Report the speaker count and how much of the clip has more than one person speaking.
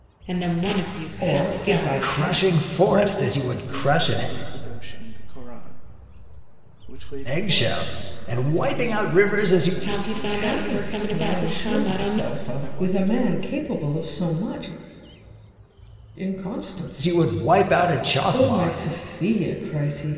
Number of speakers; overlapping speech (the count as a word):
four, about 53%